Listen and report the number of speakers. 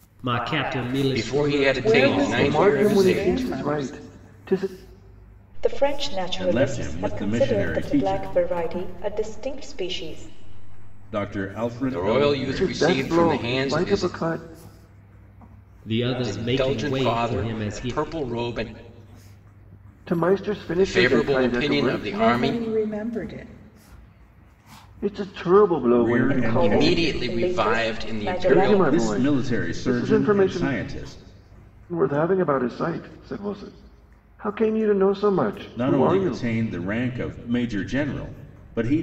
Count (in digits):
6